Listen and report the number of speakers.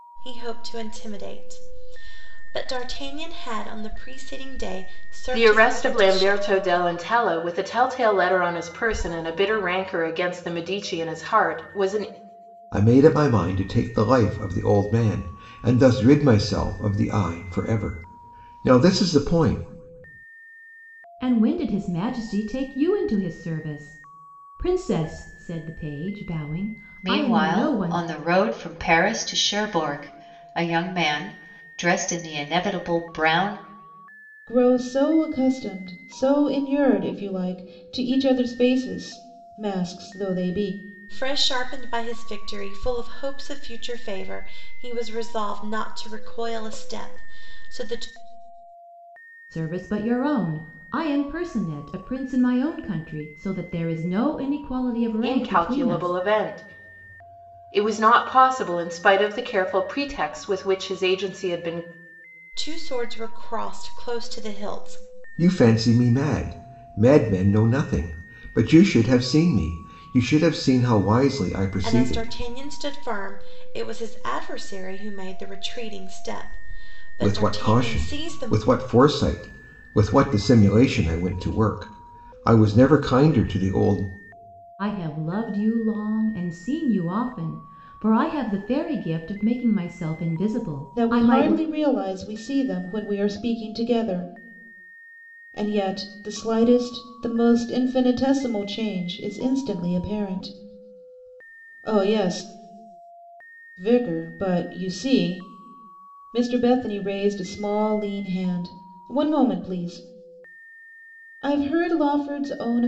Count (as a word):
six